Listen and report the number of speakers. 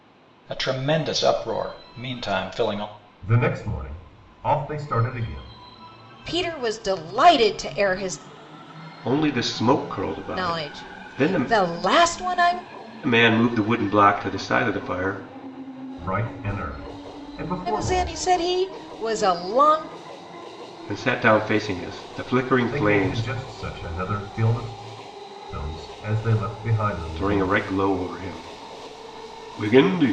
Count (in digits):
4